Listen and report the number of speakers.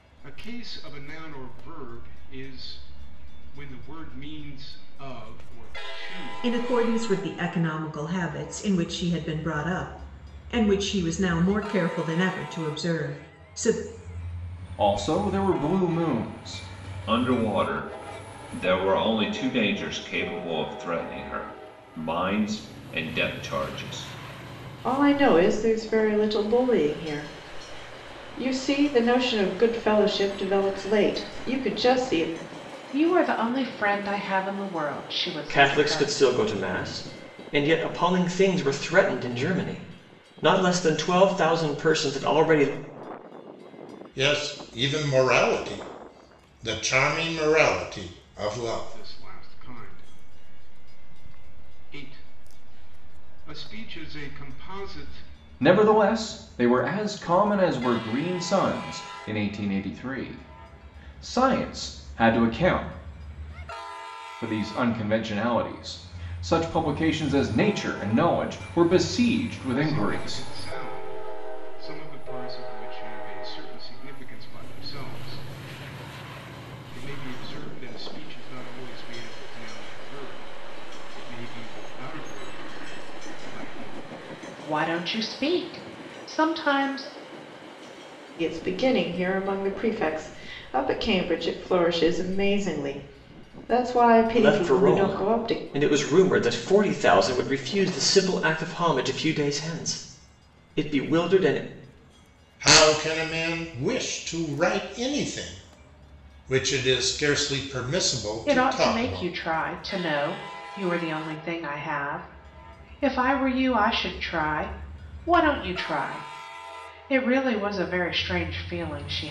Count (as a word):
eight